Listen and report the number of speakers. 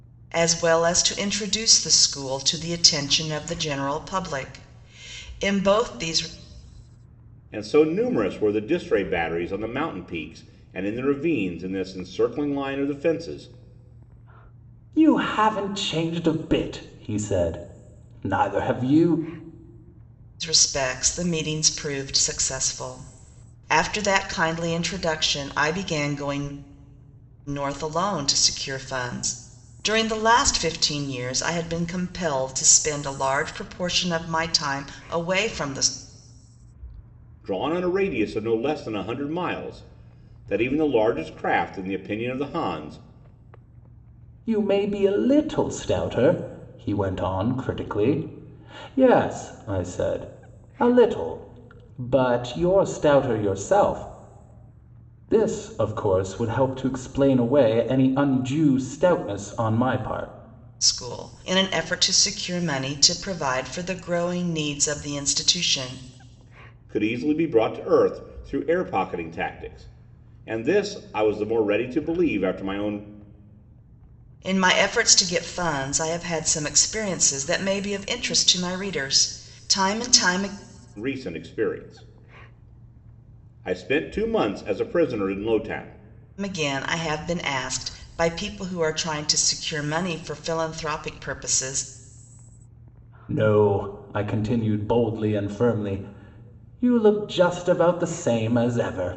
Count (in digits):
3